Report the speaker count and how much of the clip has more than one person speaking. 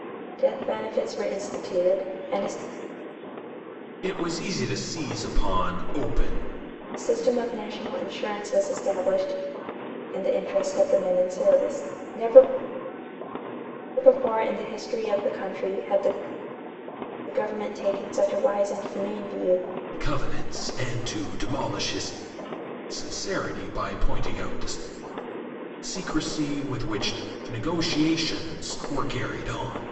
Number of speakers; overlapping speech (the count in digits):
2, no overlap